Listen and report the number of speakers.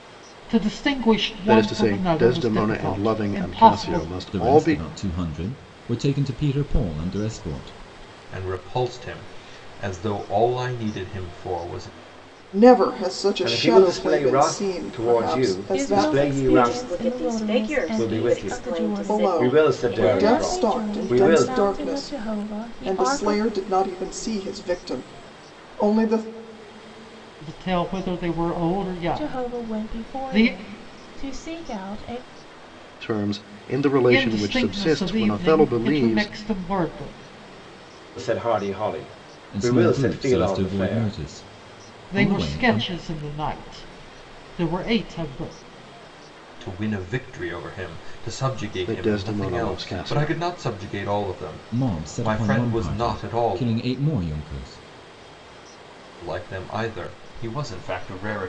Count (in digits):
8